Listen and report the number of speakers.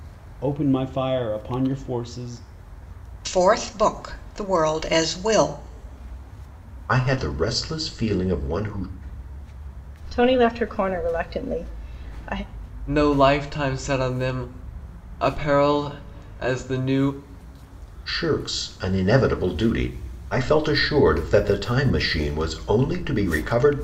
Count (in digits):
5